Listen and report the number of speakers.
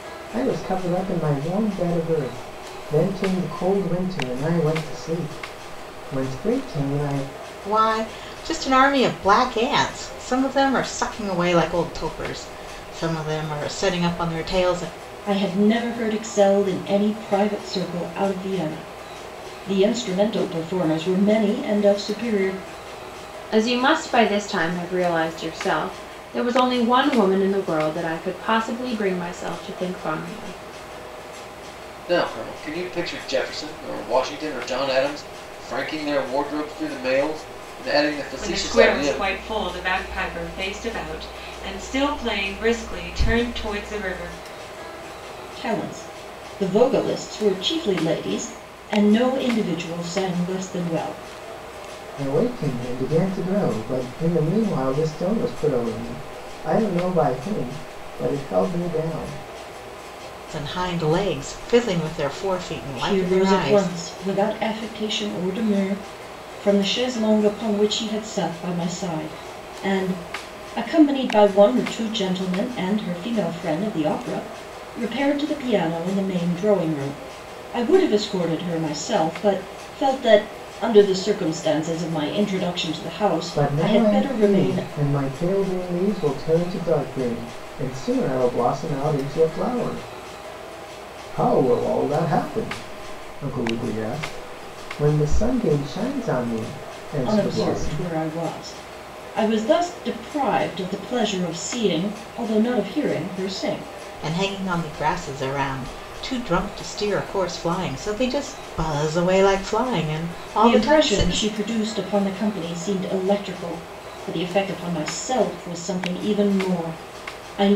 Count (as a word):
six